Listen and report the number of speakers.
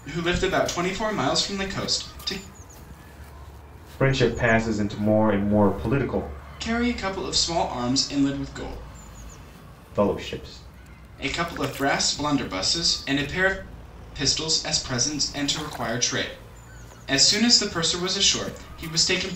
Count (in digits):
2